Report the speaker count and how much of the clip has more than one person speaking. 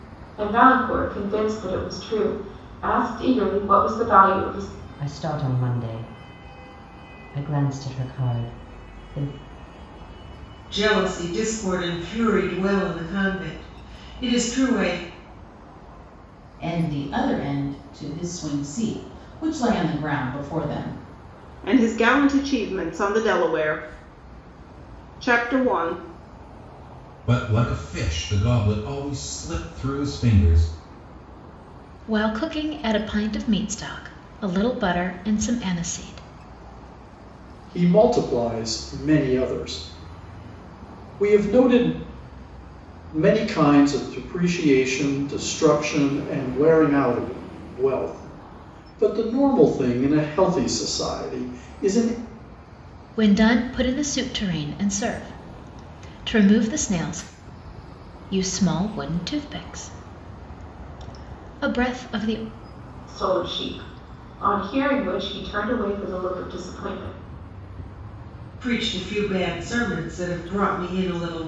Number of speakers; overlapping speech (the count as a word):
eight, no overlap